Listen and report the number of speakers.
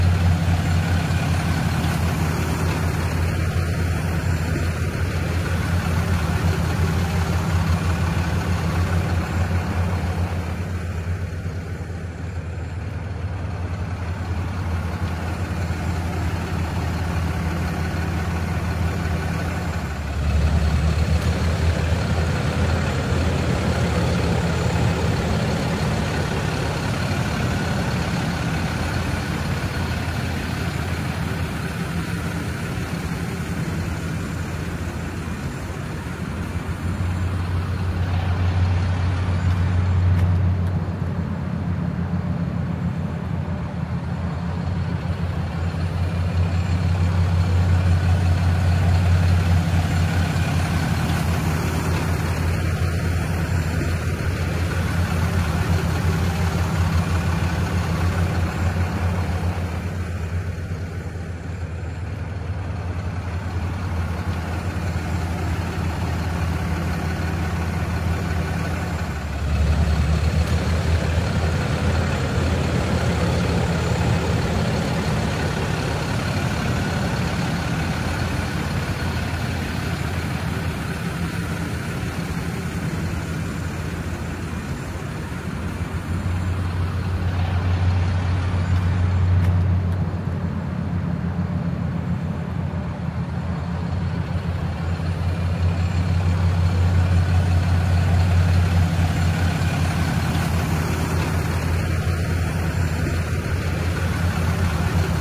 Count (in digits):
0